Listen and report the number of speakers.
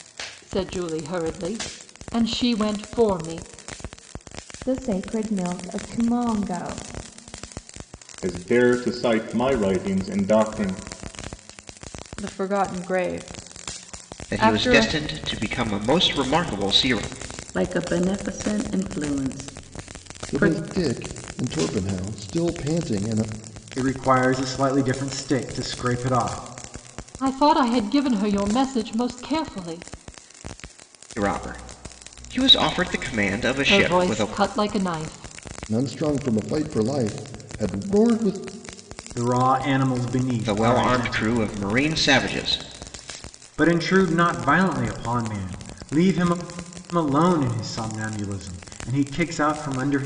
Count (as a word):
eight